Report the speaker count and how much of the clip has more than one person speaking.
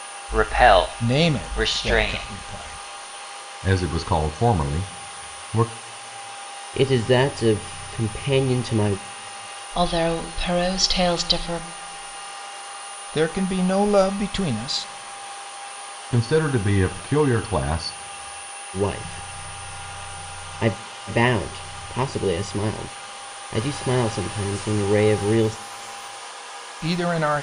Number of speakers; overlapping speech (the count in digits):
5, about 5%